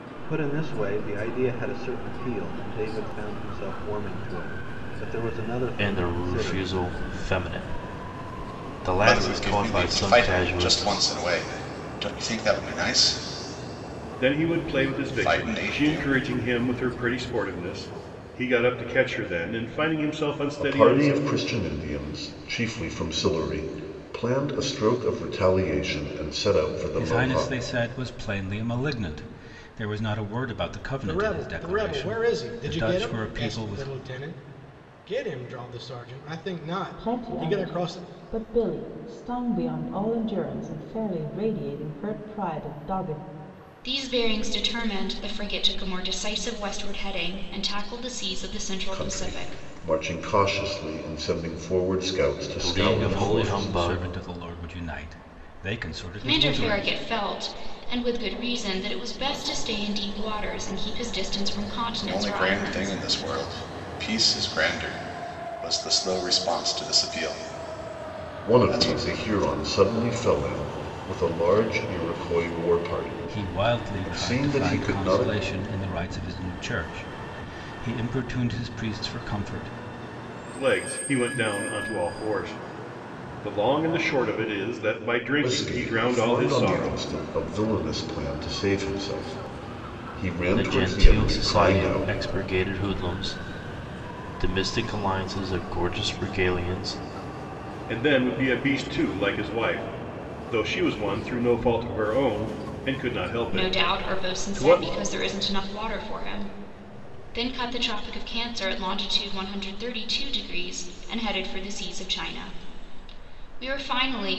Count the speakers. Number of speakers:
9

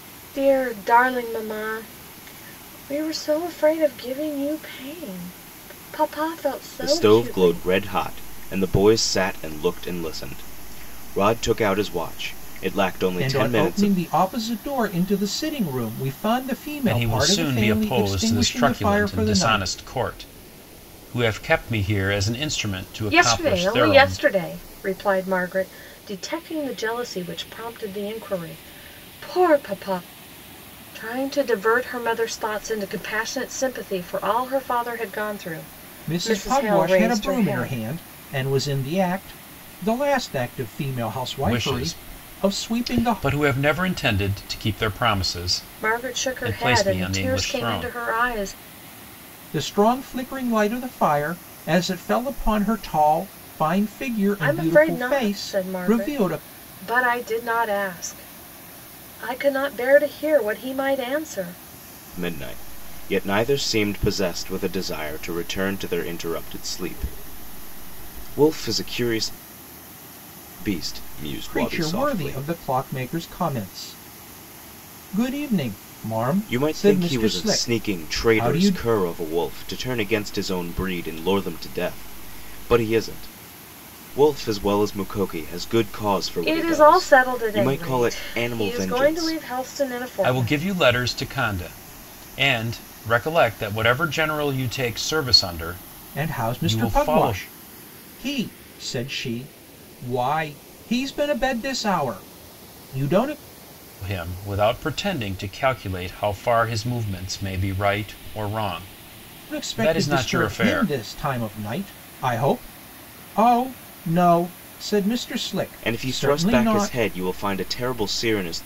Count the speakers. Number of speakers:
4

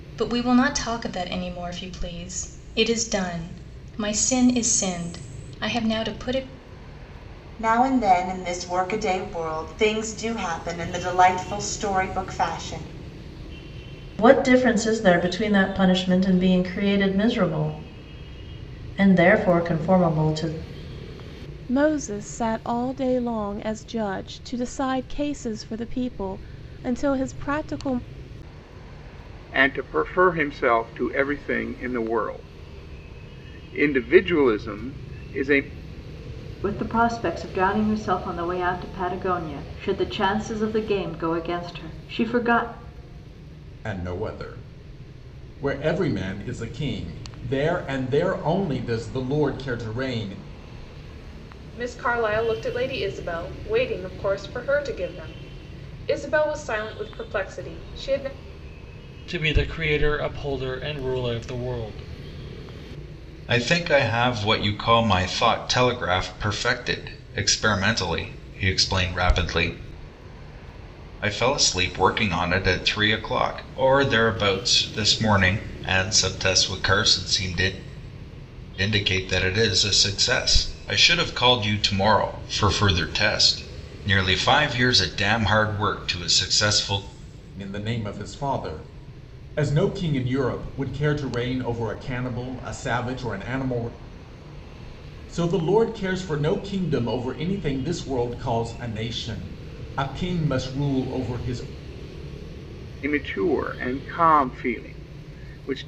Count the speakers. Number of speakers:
10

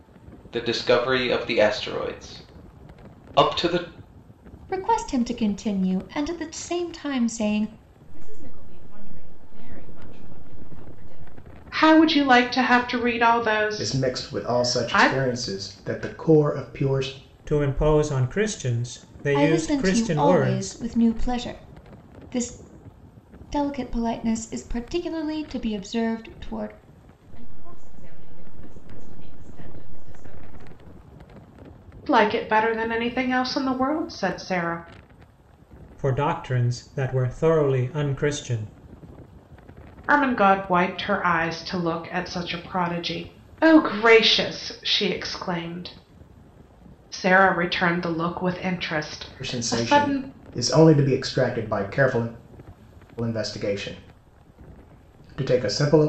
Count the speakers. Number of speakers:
6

